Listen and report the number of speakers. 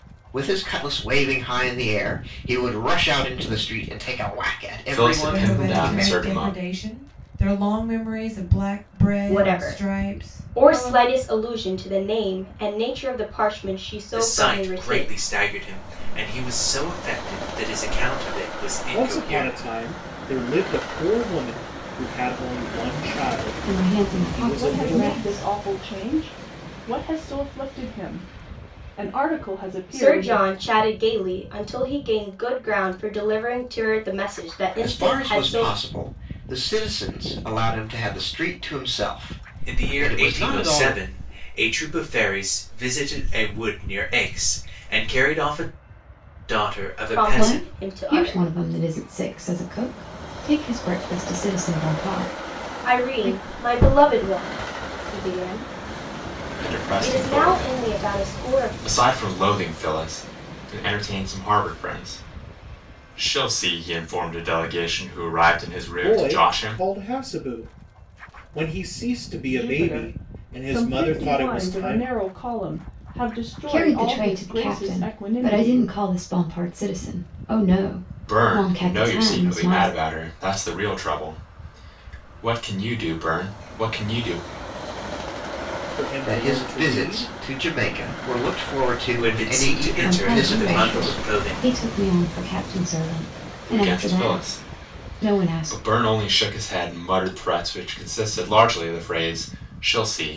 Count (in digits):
8